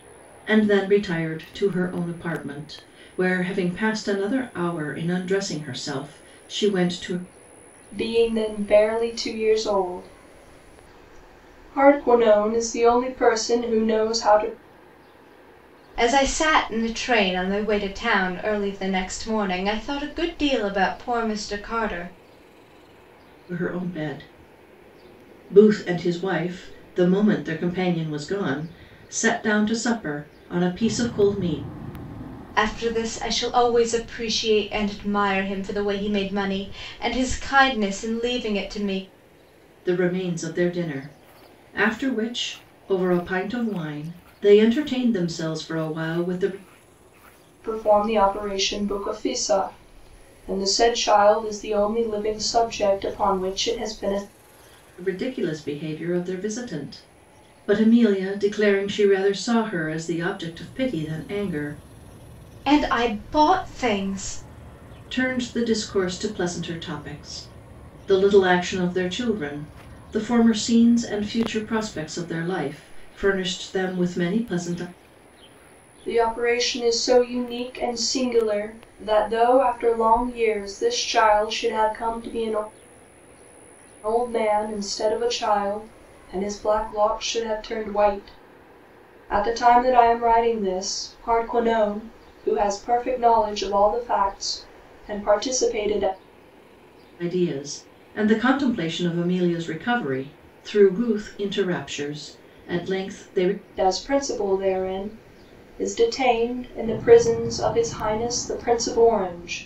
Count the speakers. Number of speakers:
three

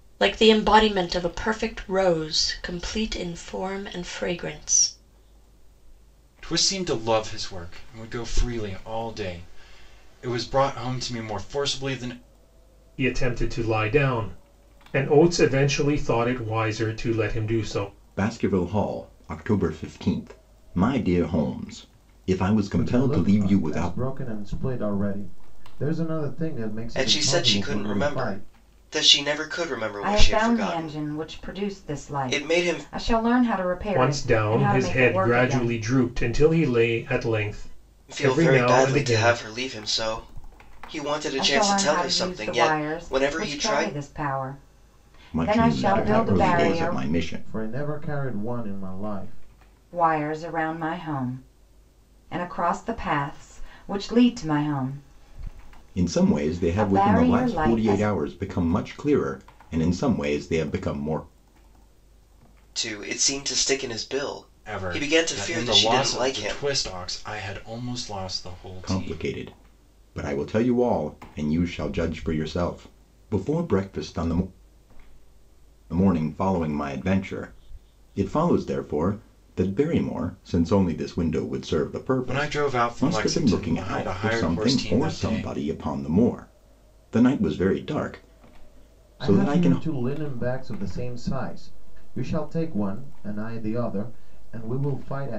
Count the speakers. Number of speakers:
seven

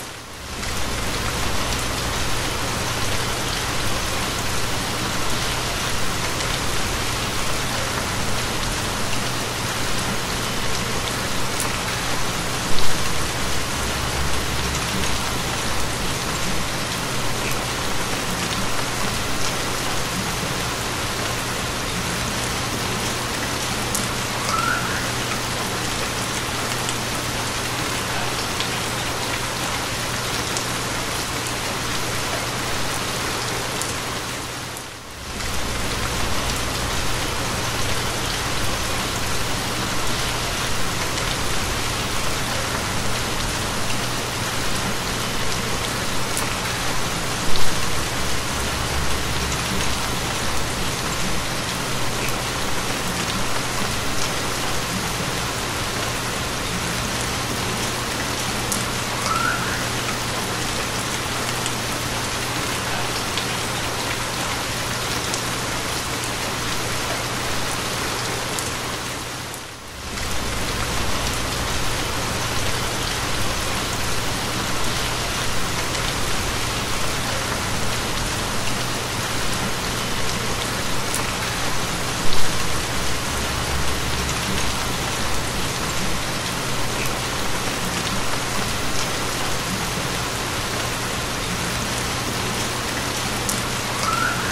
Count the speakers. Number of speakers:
zero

